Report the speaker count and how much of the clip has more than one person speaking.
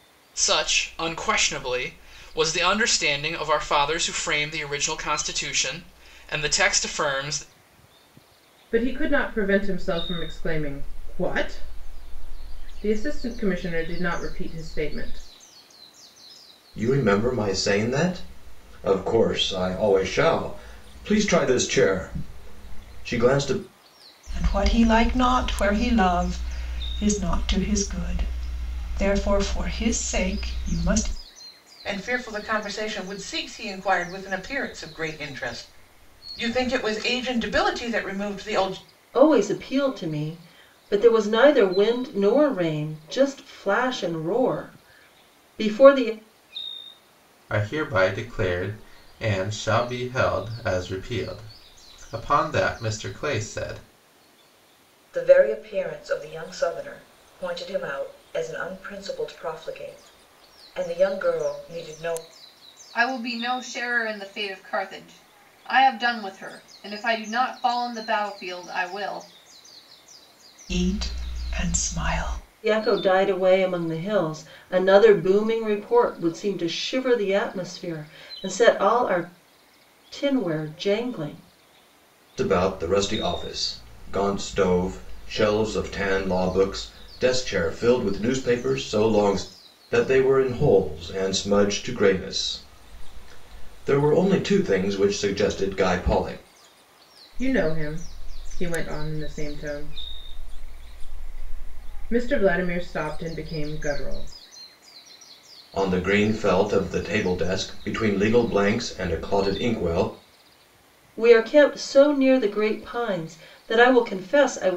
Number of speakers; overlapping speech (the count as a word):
nine, no overlap